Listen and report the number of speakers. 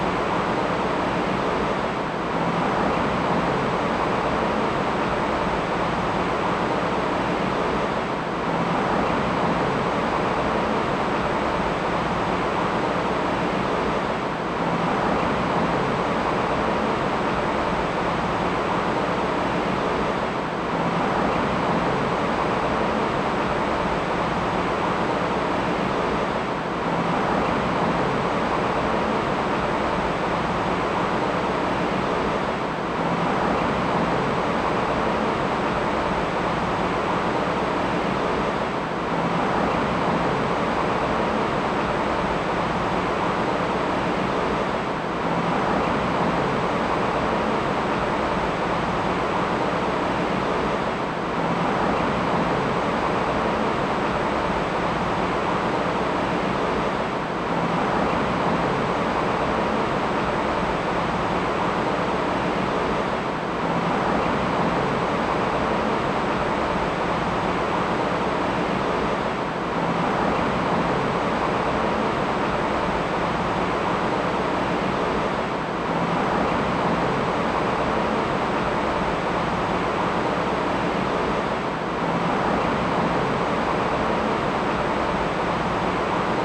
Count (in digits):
0